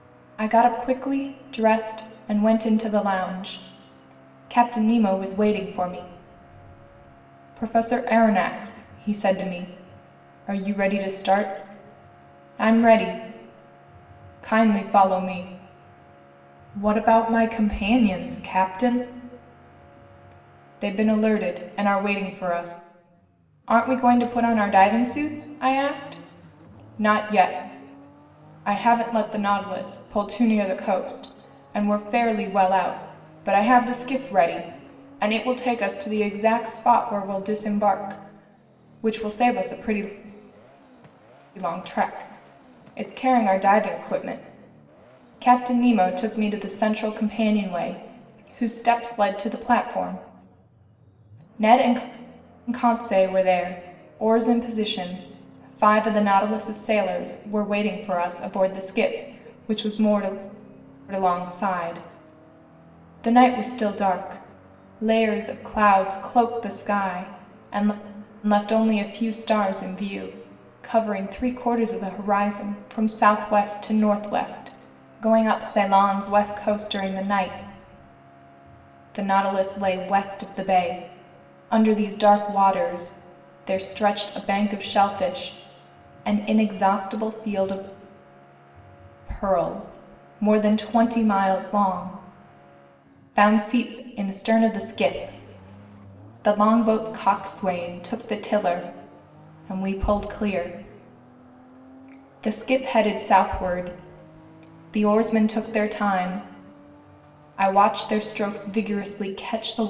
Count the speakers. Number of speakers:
one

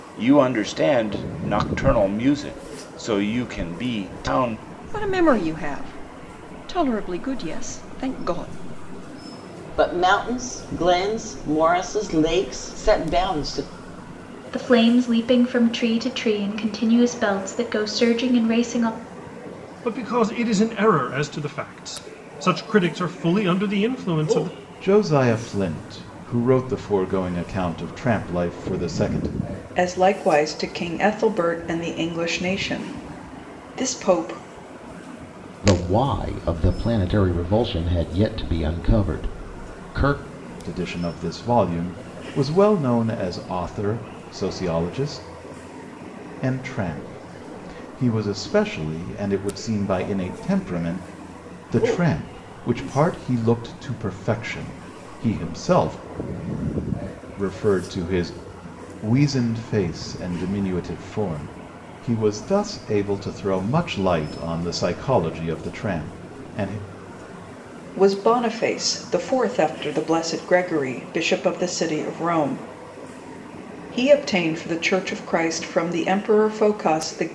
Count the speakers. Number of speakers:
eight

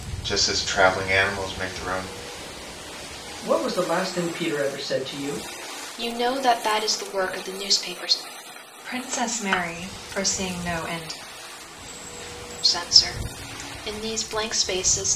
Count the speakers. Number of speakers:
four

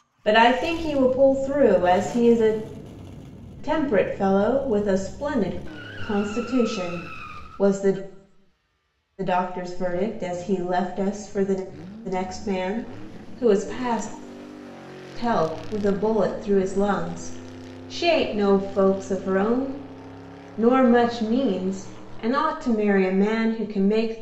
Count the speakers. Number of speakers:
one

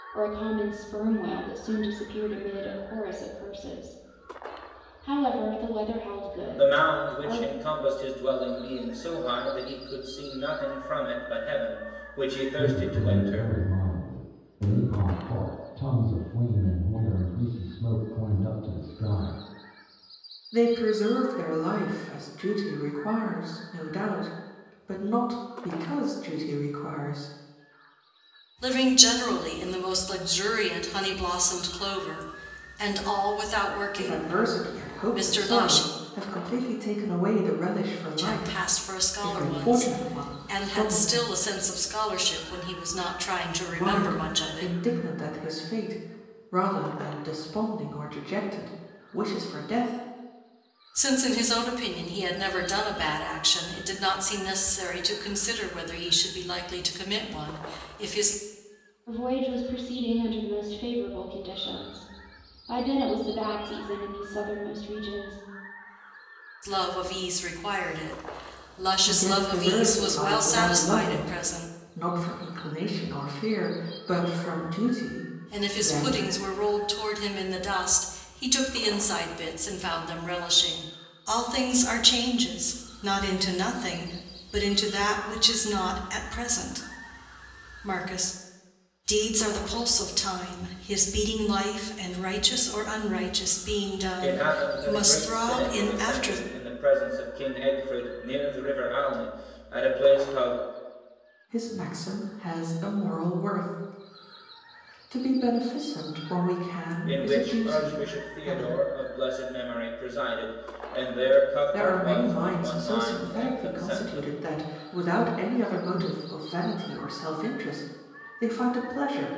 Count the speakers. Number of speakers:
five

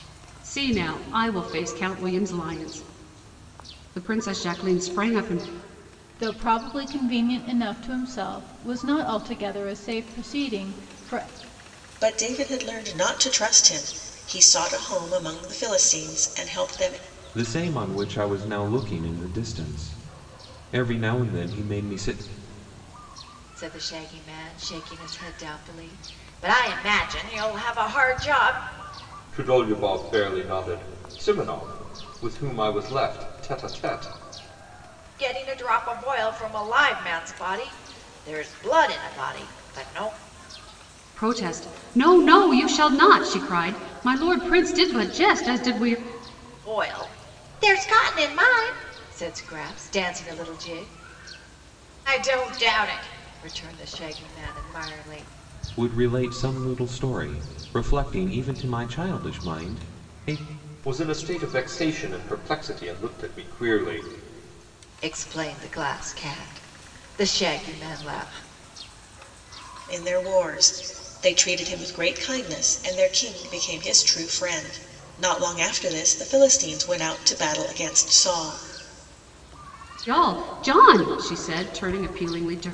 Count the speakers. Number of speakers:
six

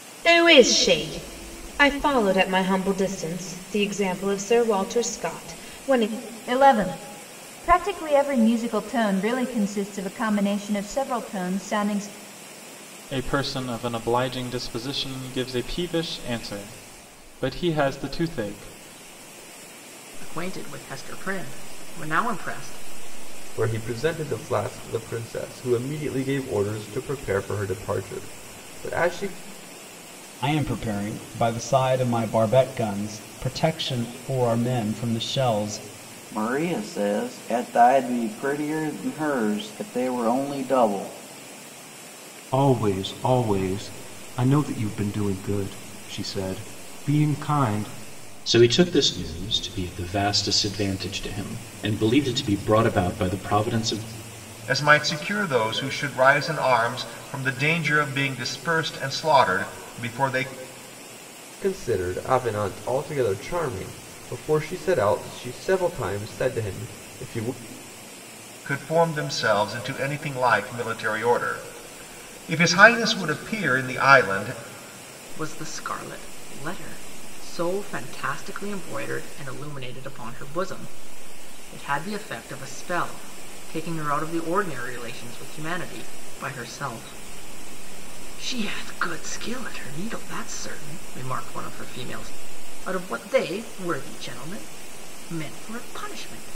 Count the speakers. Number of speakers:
ten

